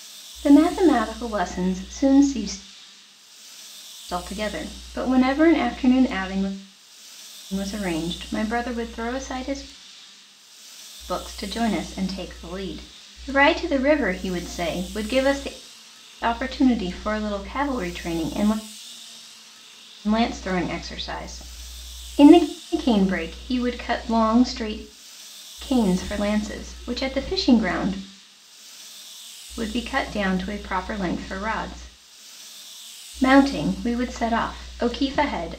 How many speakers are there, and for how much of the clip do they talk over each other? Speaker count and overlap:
one, no overlap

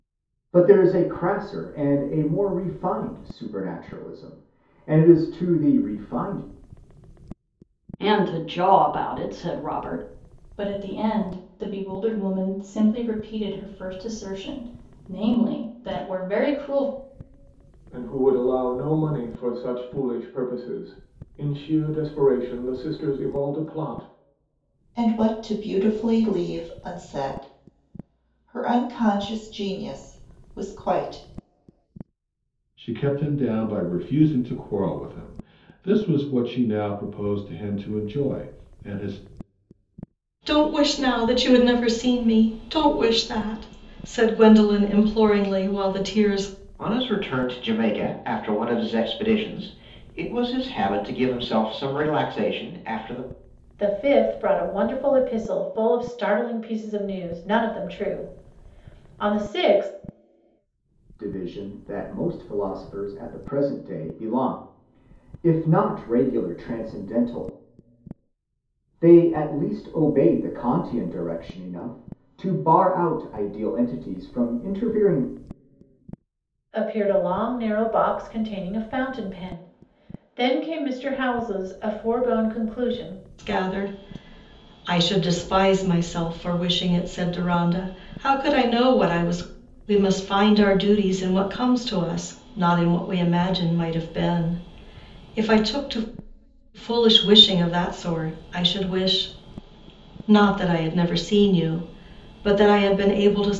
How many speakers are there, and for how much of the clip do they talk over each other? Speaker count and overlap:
nine, no overlap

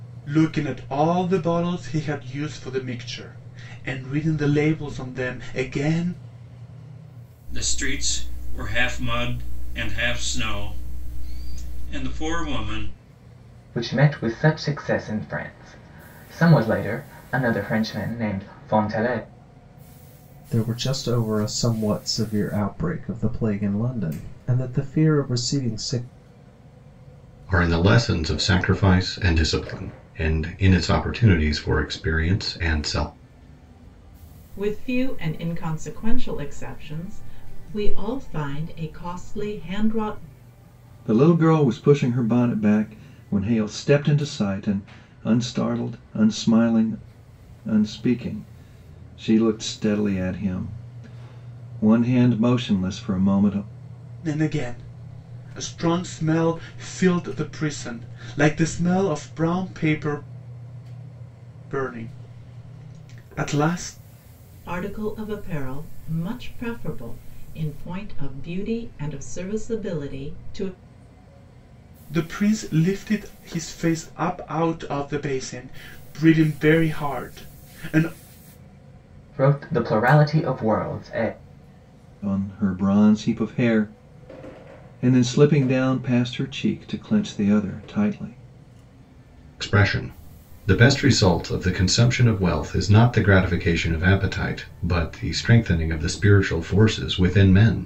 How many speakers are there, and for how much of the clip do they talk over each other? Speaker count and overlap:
seven, no overlap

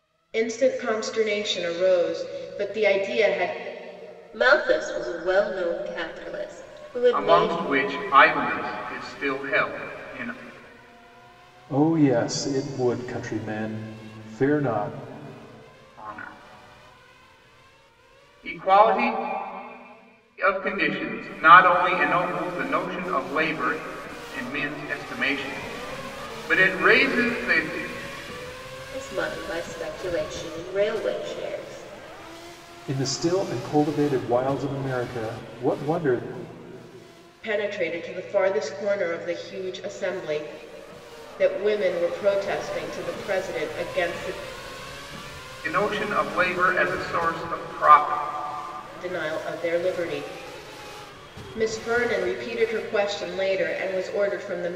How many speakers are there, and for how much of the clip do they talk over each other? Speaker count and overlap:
four, about 1%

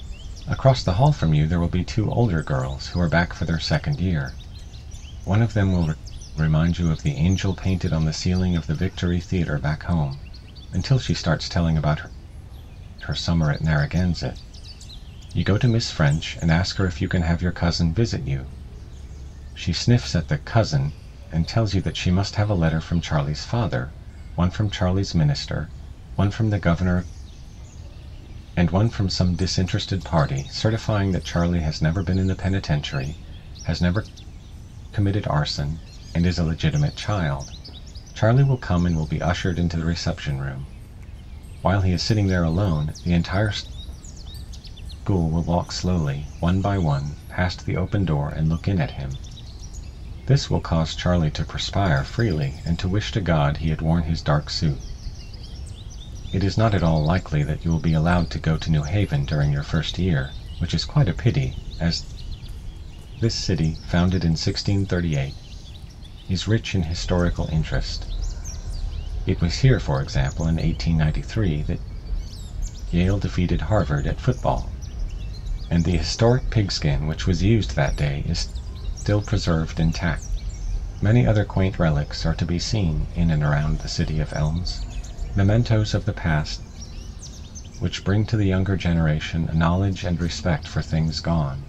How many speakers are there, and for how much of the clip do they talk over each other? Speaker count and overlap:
one, no overlap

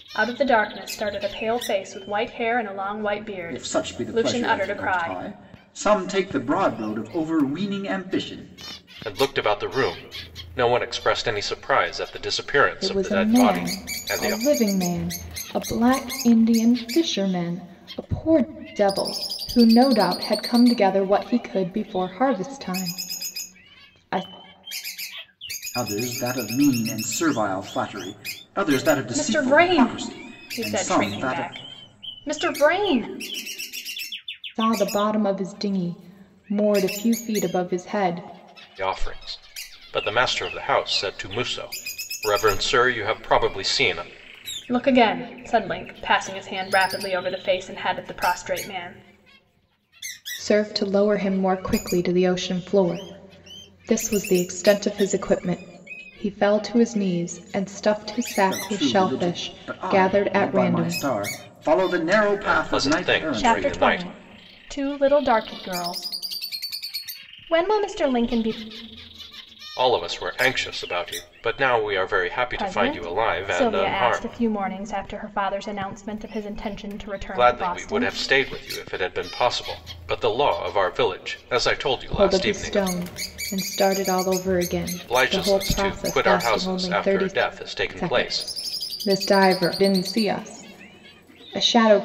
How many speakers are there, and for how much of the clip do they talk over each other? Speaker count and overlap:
four, about 18%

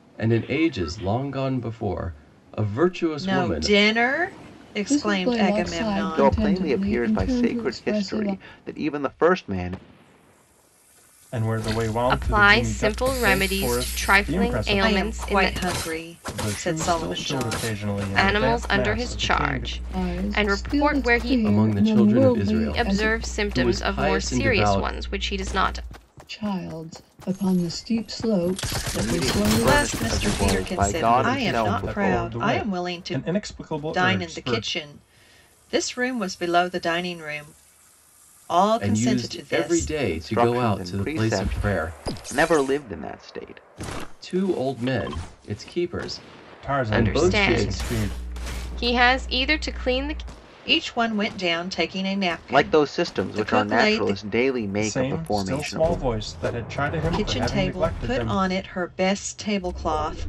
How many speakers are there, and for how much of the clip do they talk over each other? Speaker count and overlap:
six, about 50%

